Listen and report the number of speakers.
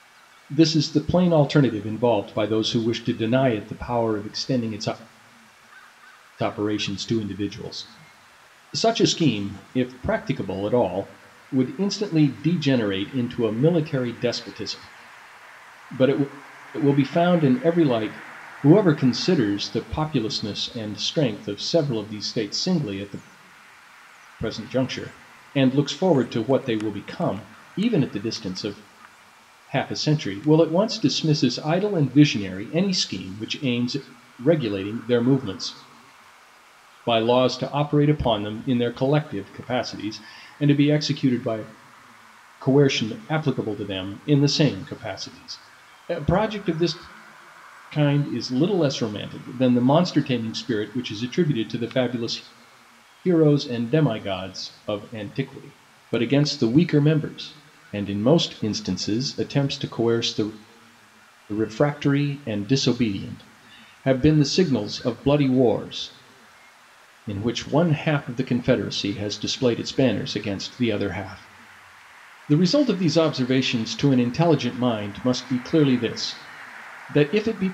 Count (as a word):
one